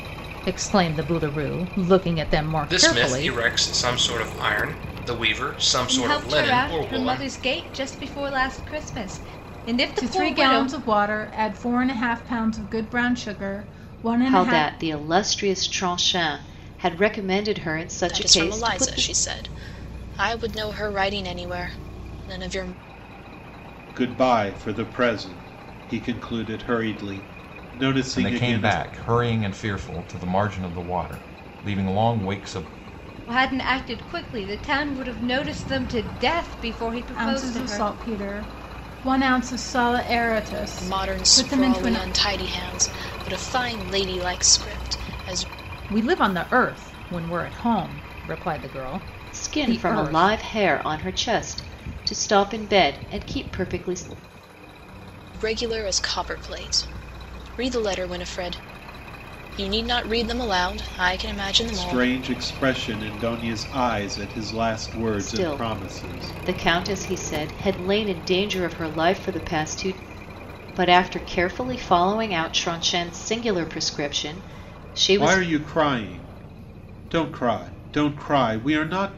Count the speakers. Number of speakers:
eight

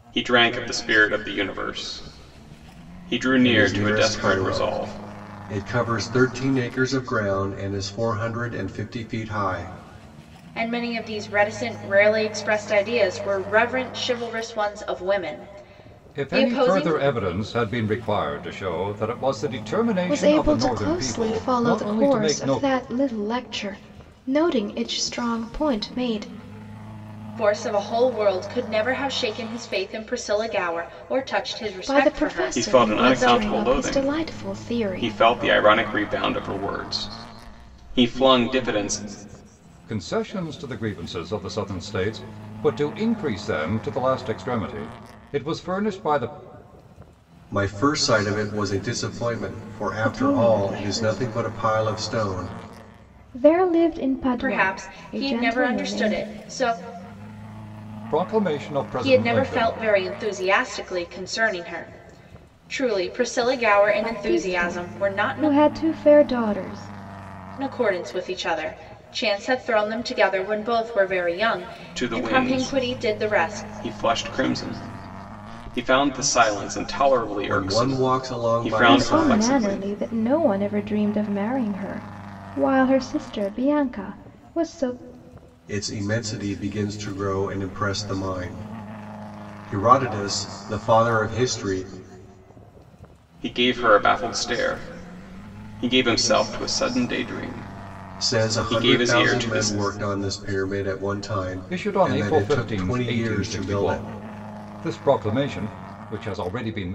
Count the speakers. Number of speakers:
five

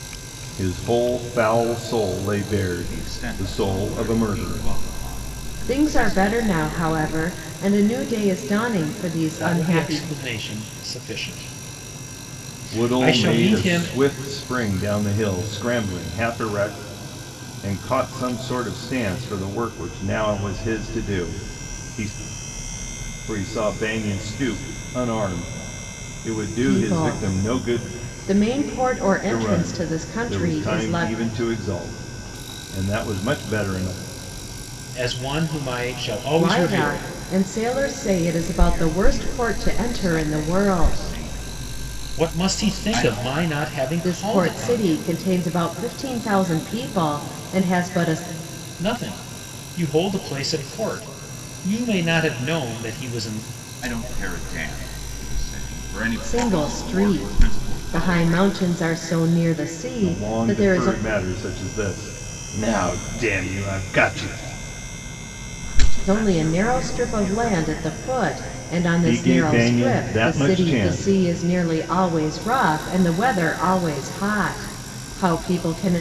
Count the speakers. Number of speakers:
four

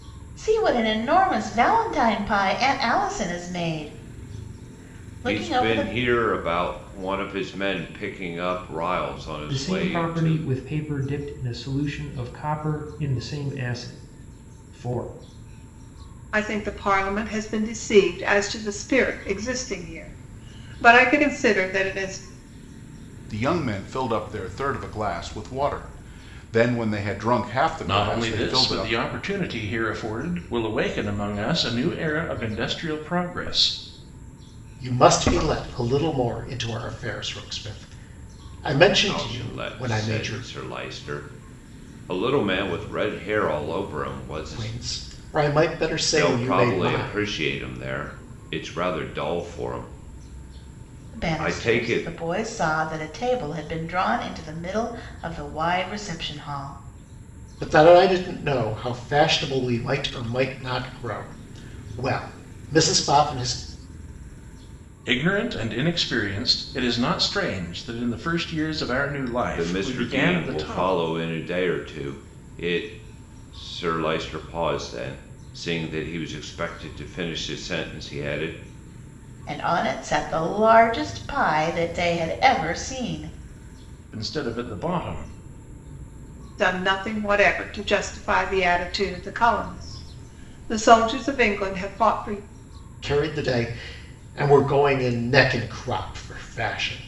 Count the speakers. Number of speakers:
seven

